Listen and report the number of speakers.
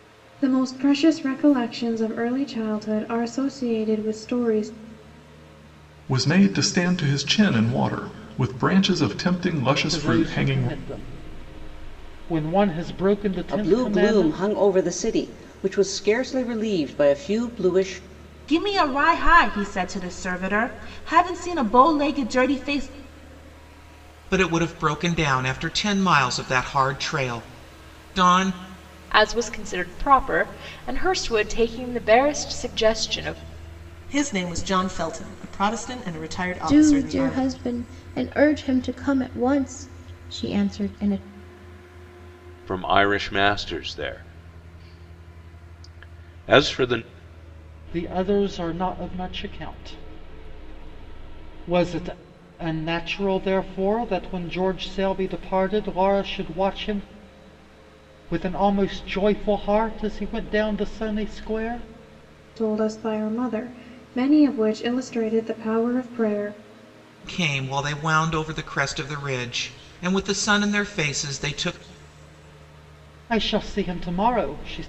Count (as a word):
ten